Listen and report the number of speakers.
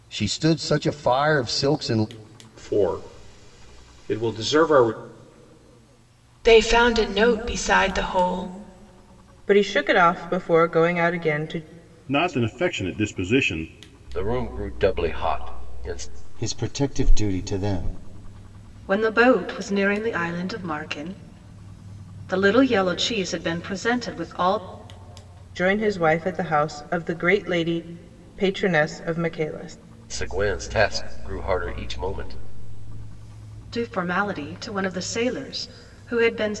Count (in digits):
8